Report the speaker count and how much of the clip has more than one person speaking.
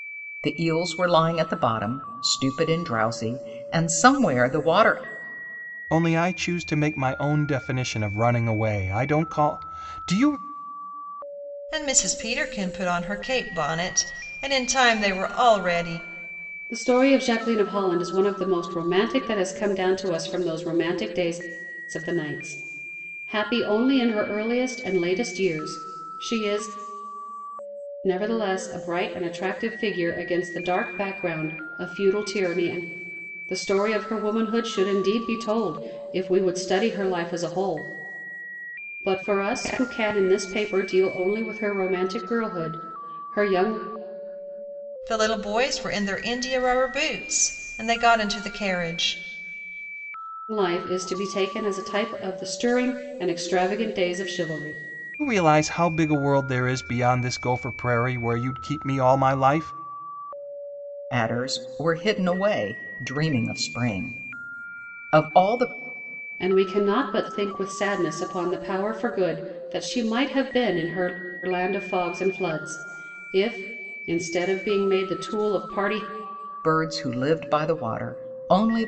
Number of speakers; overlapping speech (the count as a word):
four, no overlap